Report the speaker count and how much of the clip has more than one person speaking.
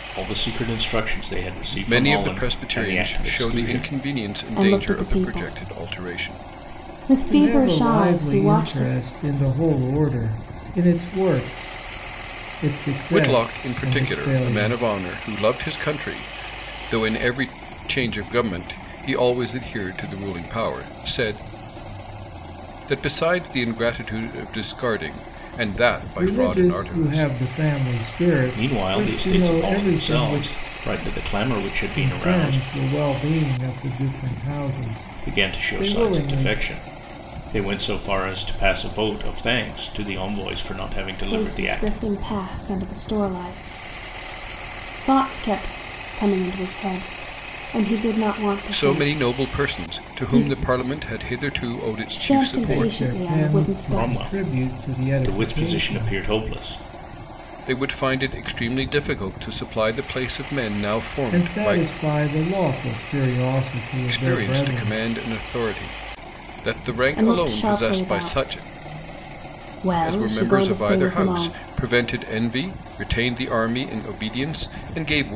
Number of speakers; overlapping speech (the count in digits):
4, about 32%